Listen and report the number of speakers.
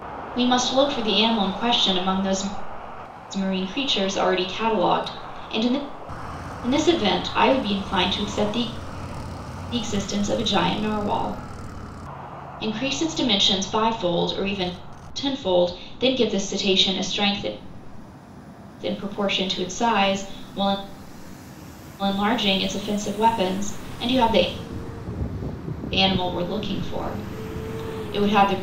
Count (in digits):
1